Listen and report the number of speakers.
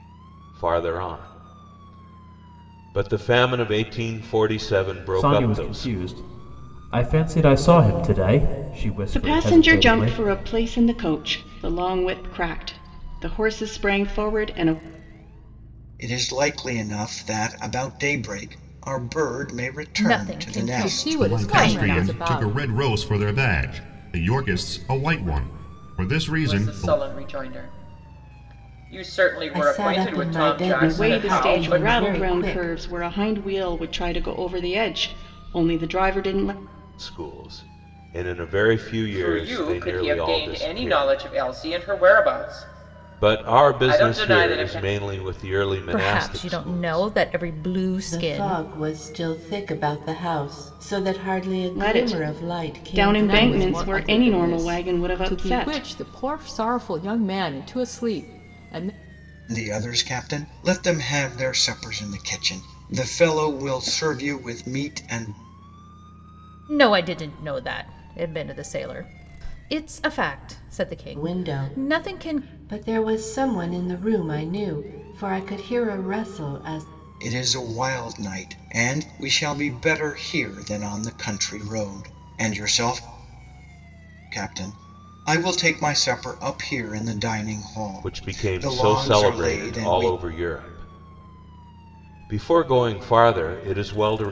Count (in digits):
9